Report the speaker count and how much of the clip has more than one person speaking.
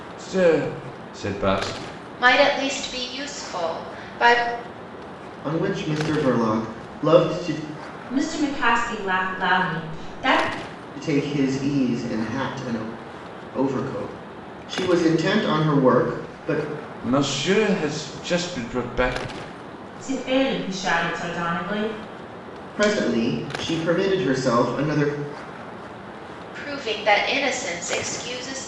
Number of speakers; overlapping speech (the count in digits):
4, no overlap